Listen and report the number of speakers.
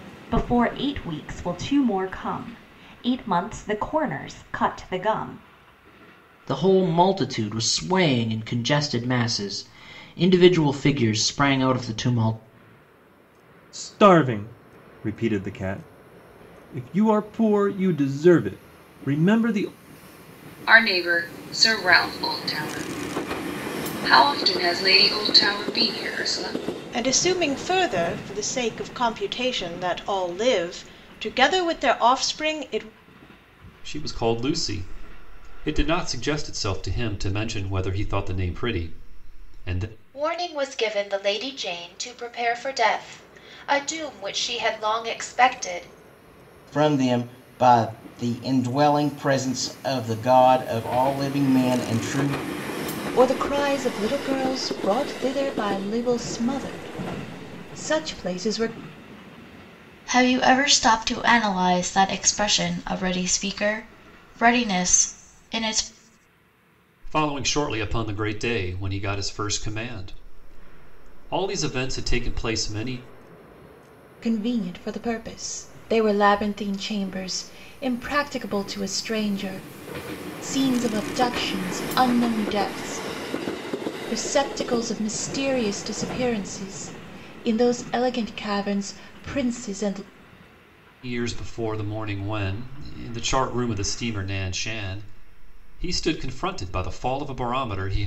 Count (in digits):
10